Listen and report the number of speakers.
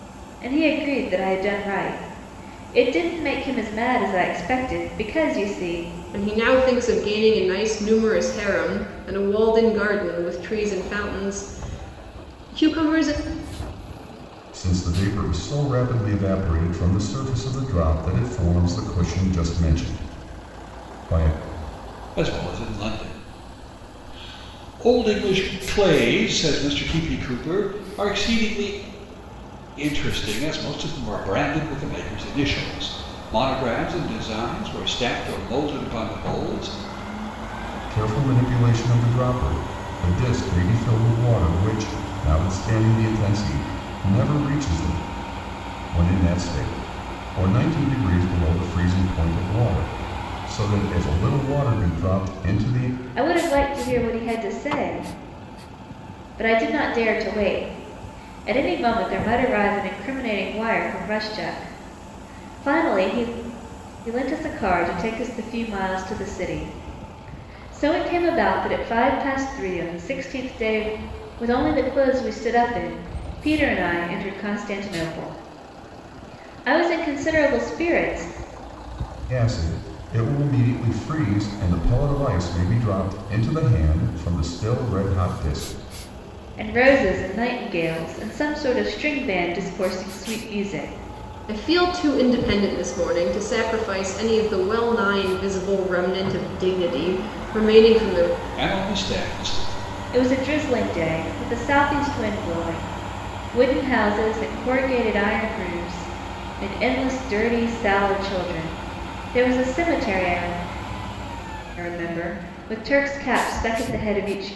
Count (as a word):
four